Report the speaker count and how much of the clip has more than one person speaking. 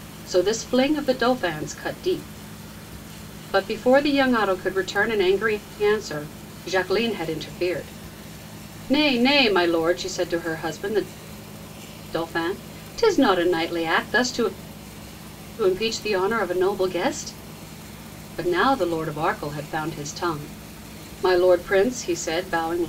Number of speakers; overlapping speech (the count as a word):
one, no overlap